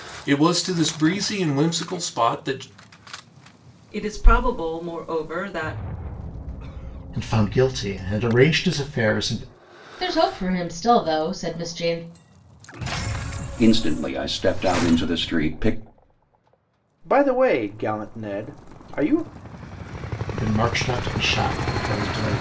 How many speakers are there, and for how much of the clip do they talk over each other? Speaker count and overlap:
six, no overlap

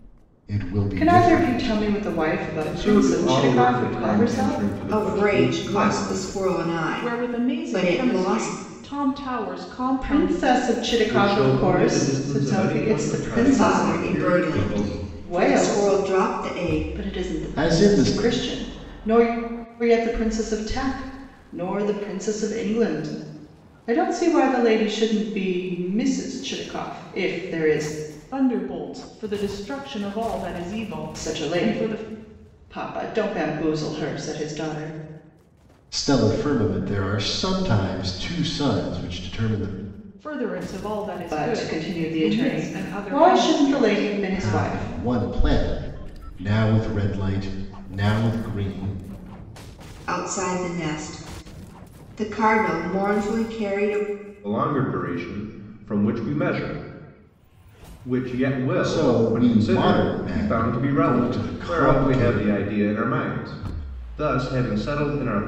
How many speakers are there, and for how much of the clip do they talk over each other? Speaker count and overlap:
five, about 34%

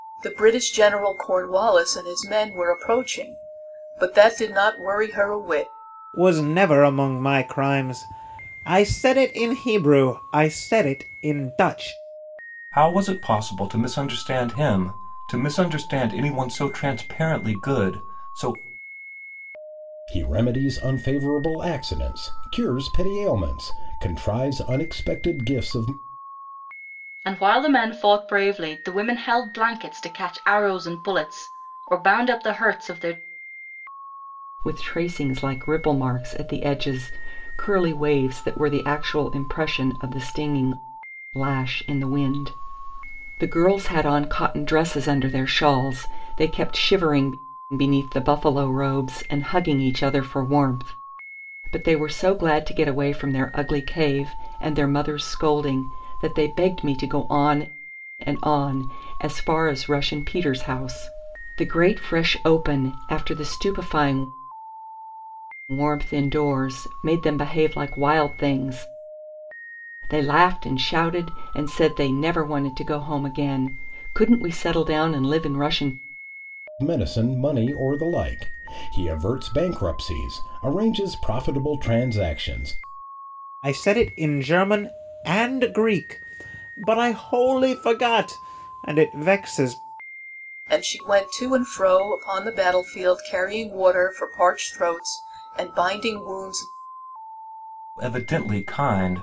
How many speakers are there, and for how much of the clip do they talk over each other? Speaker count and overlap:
six, no overlap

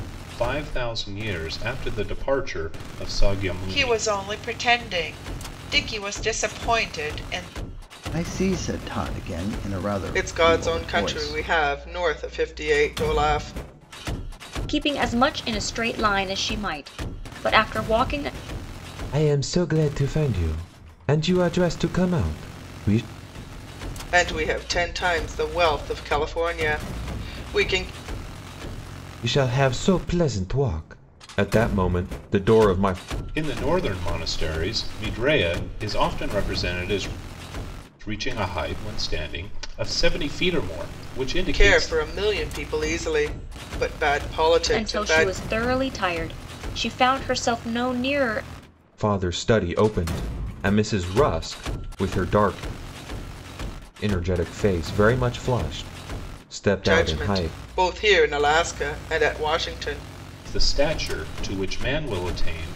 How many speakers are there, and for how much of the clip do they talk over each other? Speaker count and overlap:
six, about 6%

